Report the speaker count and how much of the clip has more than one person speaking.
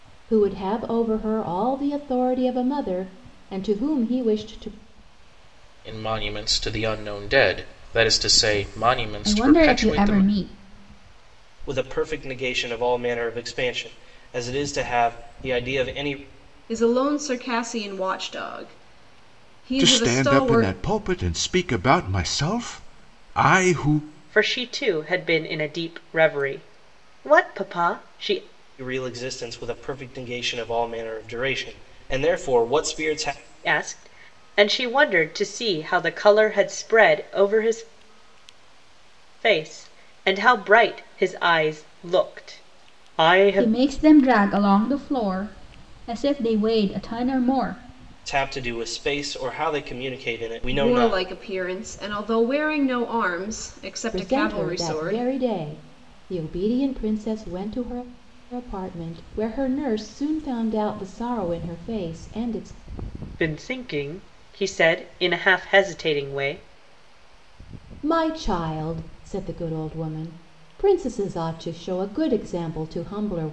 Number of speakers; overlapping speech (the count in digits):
7, about 6%